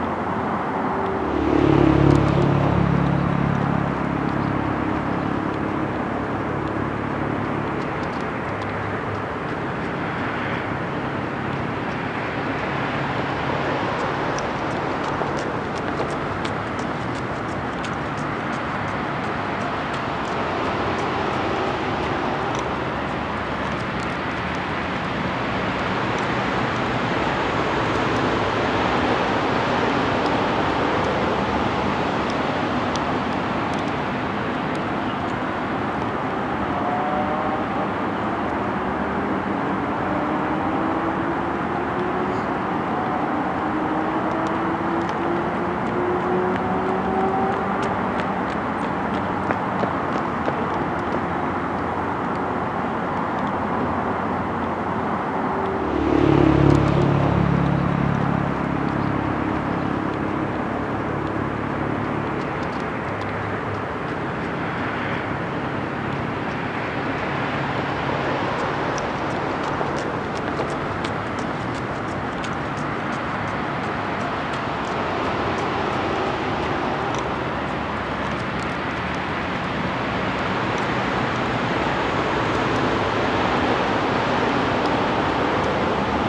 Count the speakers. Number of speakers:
0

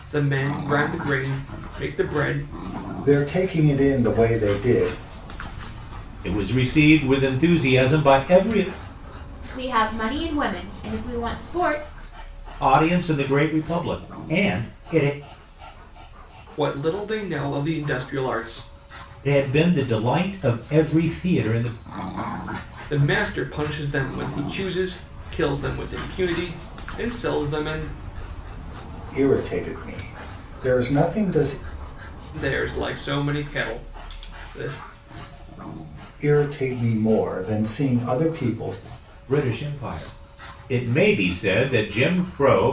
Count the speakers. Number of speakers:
4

